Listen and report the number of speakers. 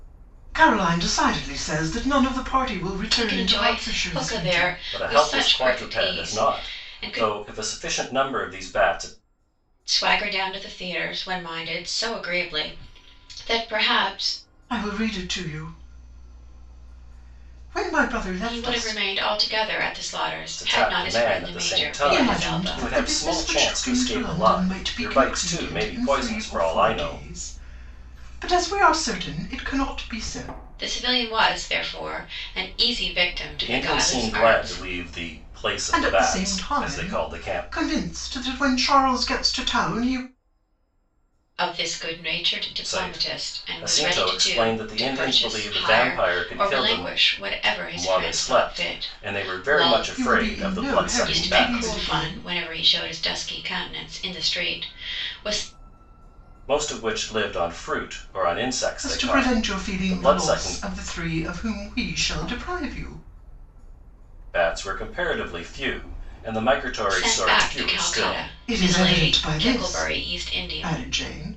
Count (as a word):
three